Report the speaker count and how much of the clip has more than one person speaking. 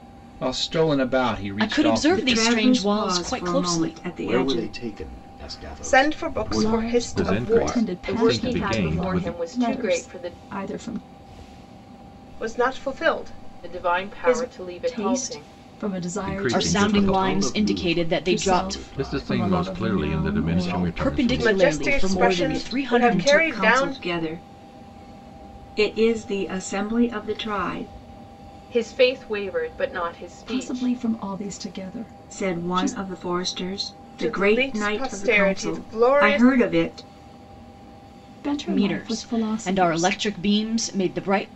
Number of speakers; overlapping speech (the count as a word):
eight, about 53%